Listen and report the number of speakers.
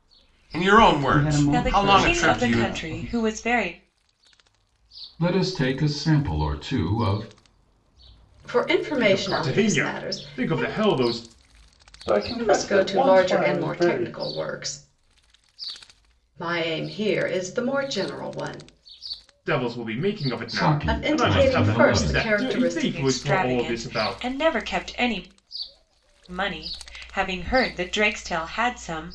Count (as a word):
seven